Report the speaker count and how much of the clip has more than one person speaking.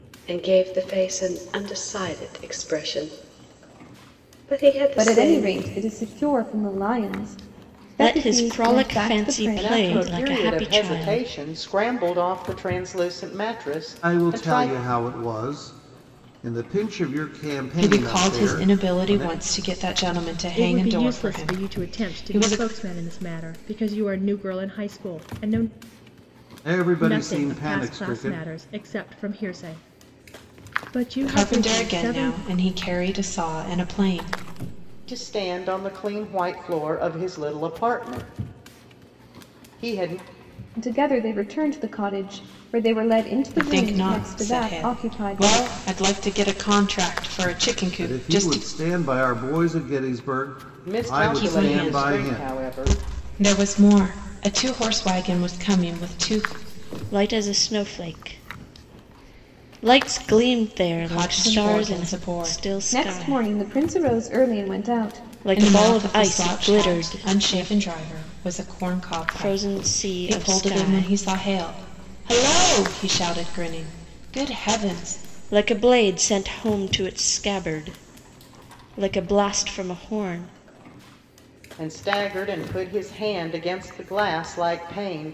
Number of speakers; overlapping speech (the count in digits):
7, about 29%